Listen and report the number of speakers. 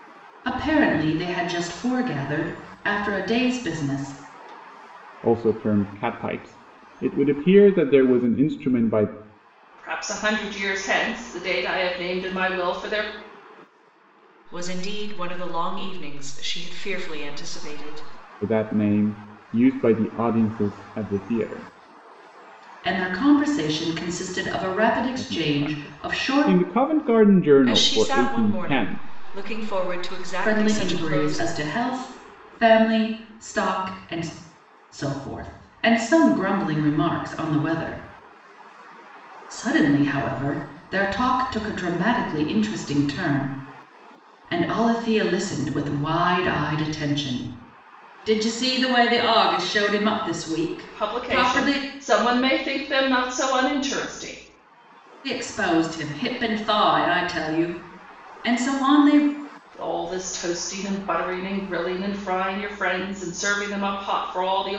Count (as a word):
four